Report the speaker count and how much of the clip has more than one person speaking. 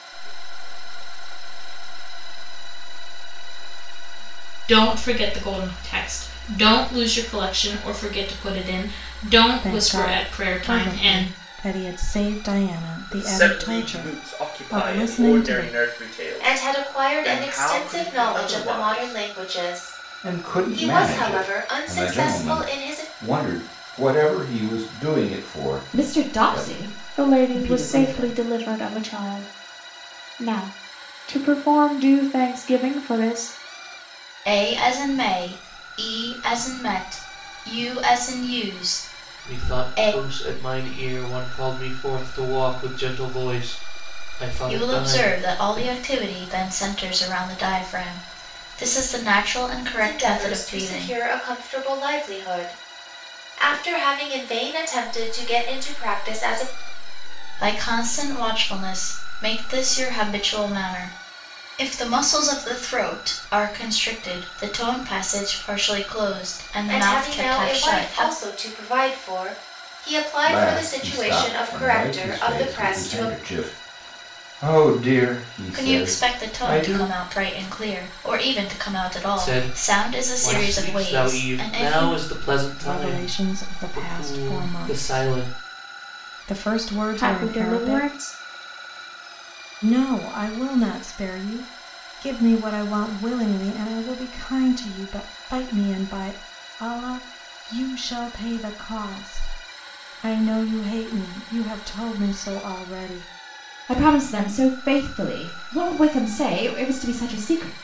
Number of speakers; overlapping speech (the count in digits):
10, about 31%